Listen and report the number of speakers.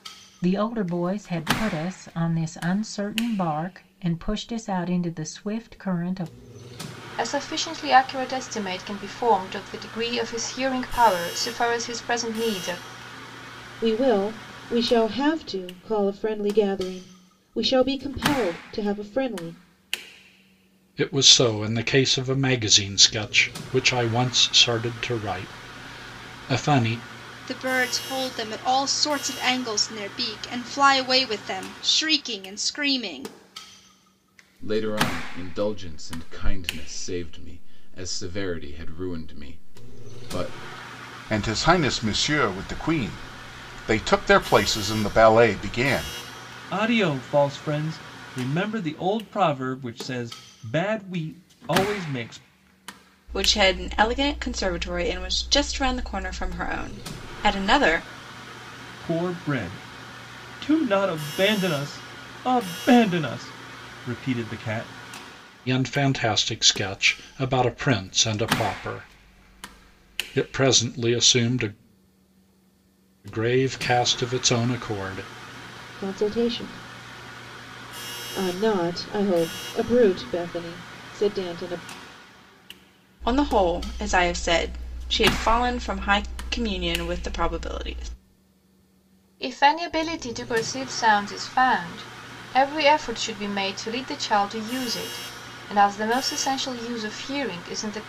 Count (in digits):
9